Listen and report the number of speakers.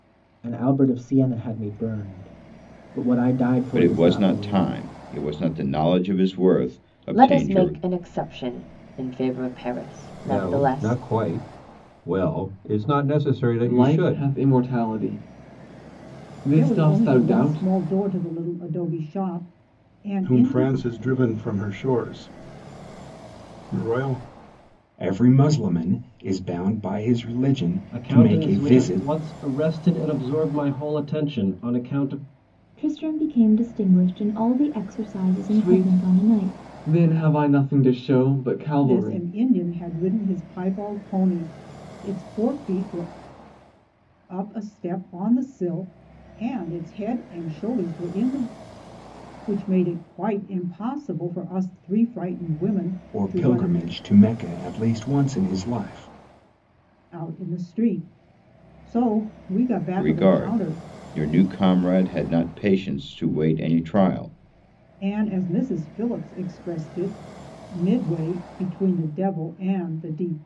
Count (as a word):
ten